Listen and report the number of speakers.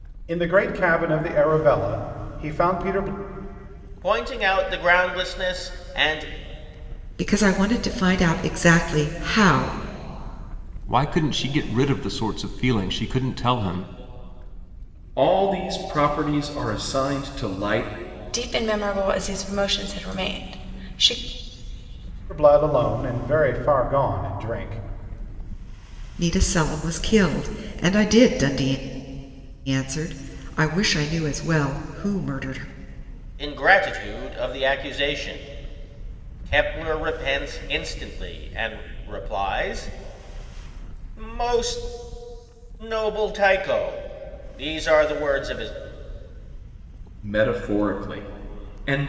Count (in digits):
6